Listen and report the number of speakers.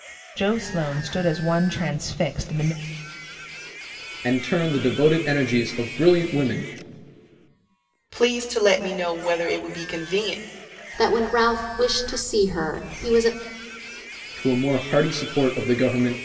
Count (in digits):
4